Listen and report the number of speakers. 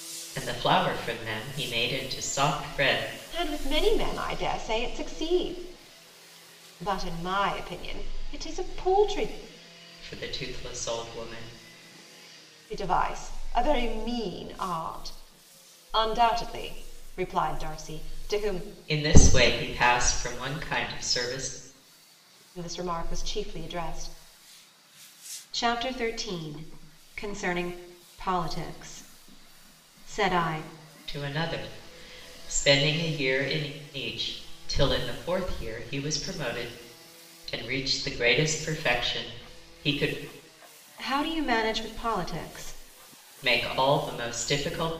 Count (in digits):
2